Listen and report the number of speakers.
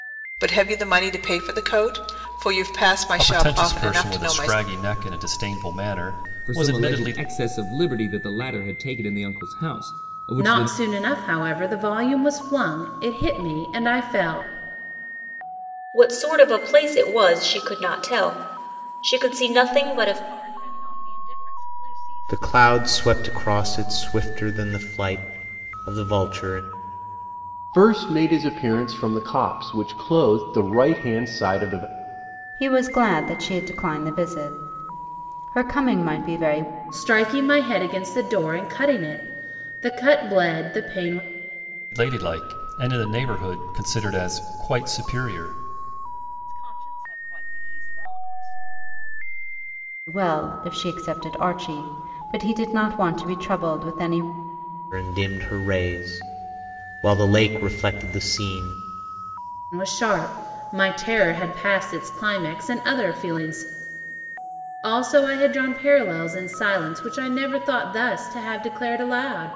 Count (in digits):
9